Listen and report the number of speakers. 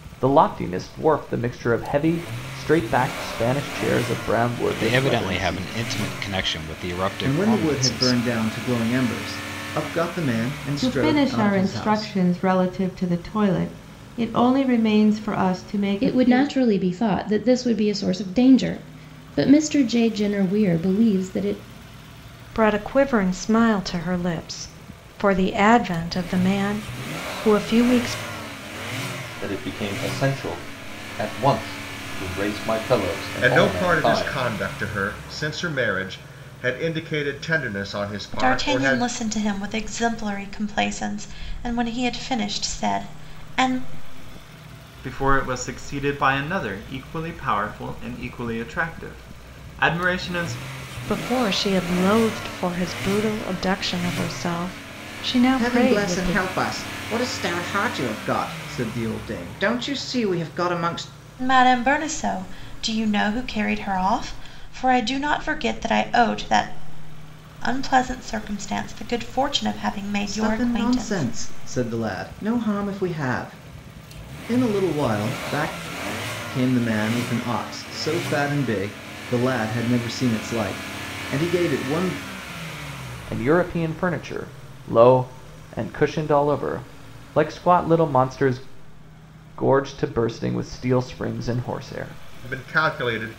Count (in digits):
10